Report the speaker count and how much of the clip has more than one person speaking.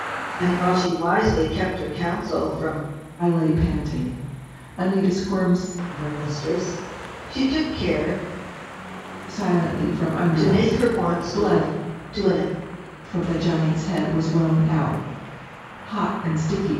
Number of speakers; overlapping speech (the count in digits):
2, about 8%